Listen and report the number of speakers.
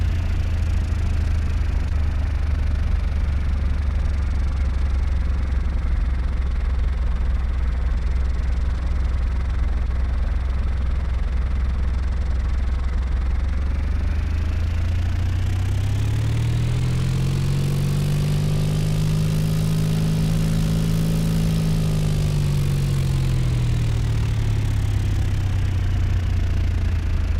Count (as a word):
zero